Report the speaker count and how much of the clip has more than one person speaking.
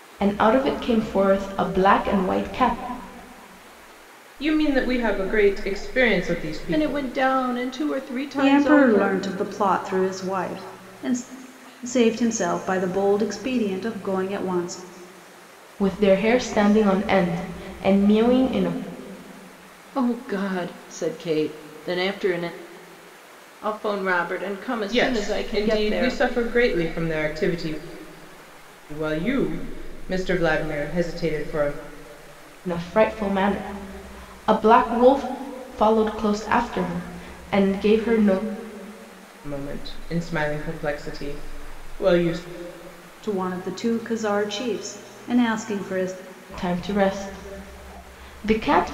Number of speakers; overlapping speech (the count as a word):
four, about 5%